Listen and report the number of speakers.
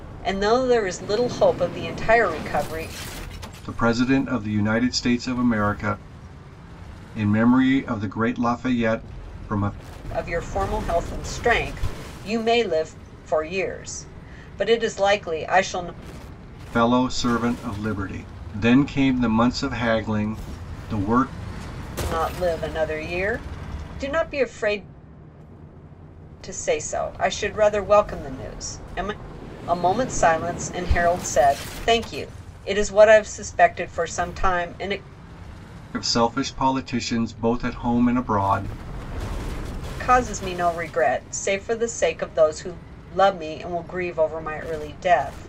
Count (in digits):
2